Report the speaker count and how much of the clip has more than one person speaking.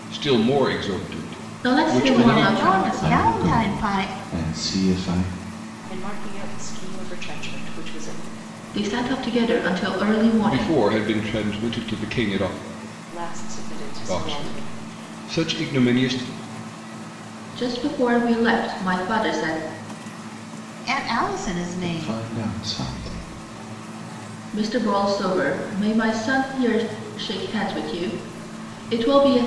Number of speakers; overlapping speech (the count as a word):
five, about 14%